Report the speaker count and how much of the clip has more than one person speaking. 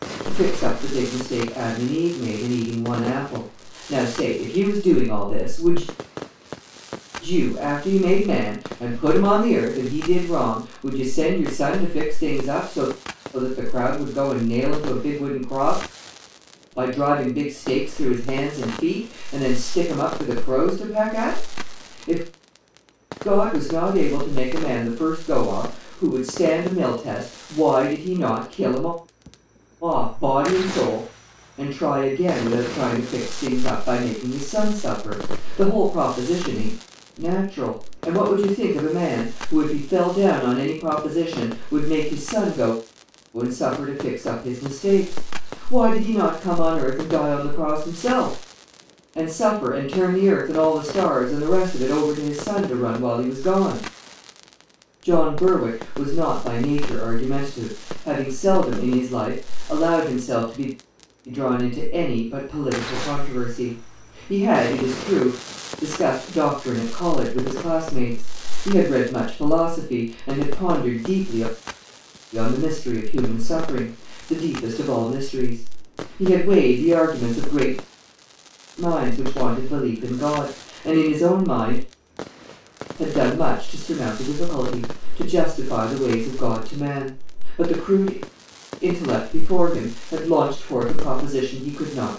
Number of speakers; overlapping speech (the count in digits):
1, no overlap